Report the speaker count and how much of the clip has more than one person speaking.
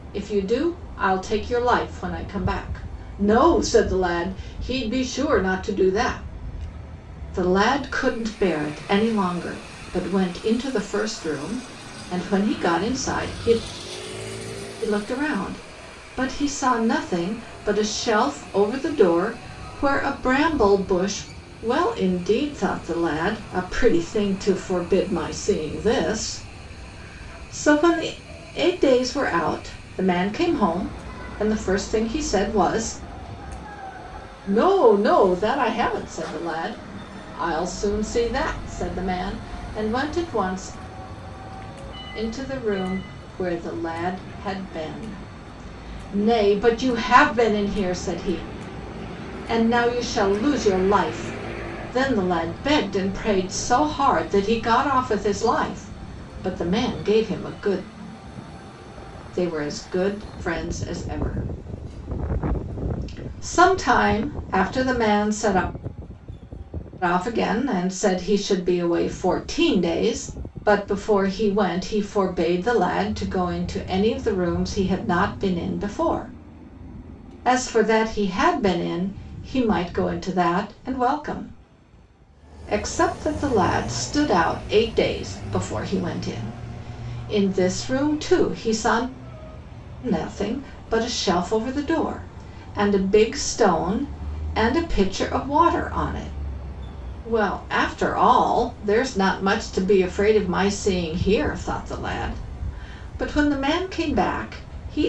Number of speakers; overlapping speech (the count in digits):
1, no overlap